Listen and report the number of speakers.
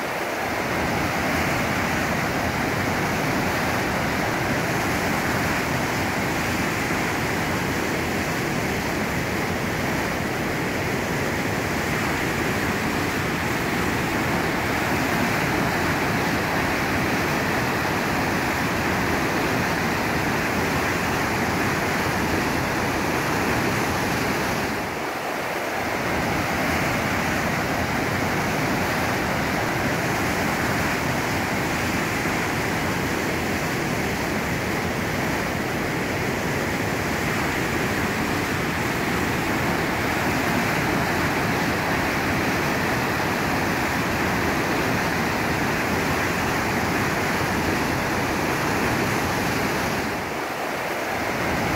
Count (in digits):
0